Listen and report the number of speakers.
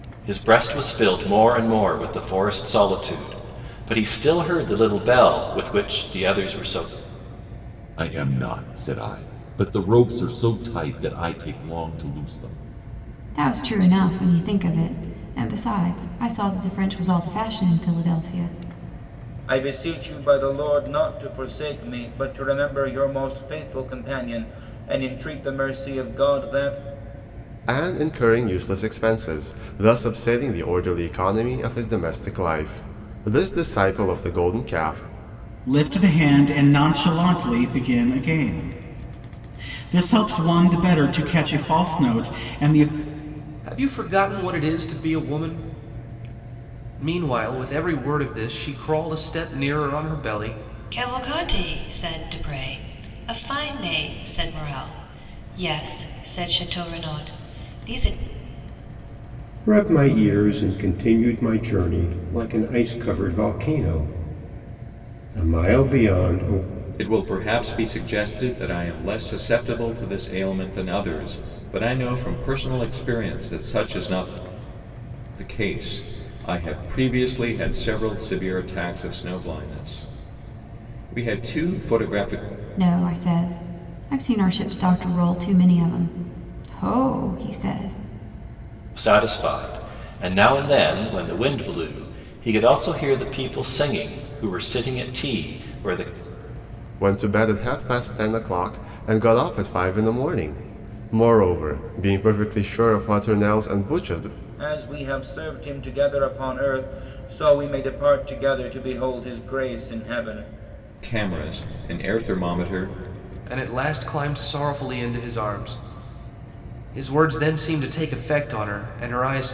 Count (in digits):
10